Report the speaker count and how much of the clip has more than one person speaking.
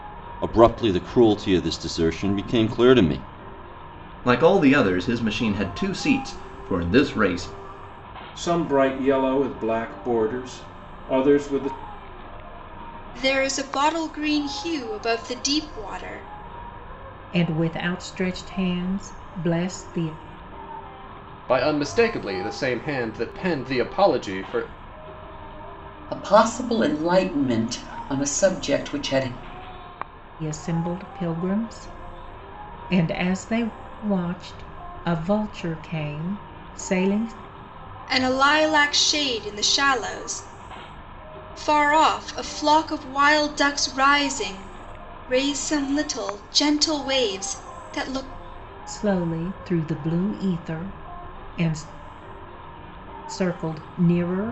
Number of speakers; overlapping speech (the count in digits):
7, no overlap